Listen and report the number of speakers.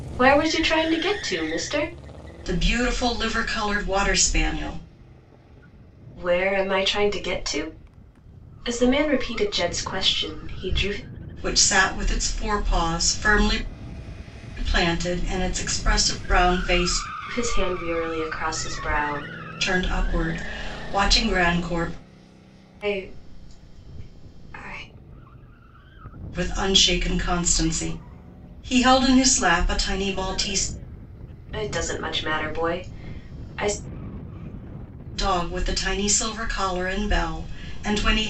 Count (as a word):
two